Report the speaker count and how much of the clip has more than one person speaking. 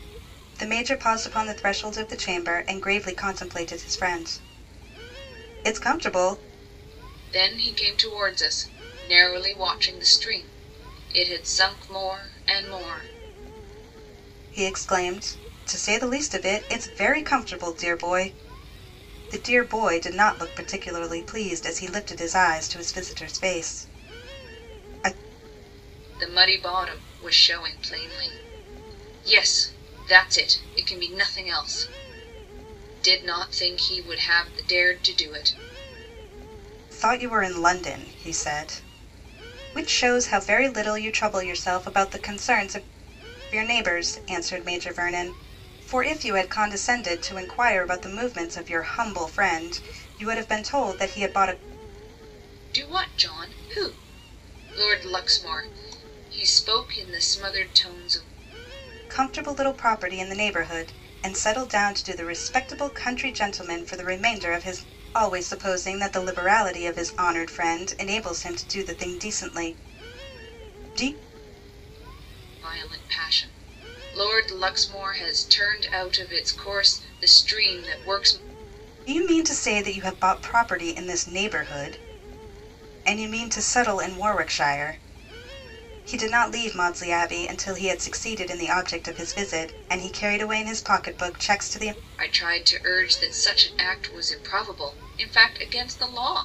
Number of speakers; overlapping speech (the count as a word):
two, no overlap